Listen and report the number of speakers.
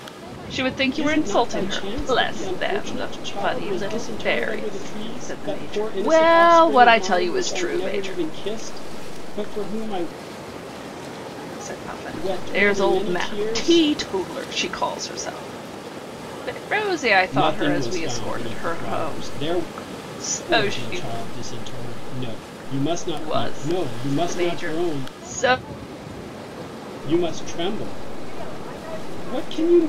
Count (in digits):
2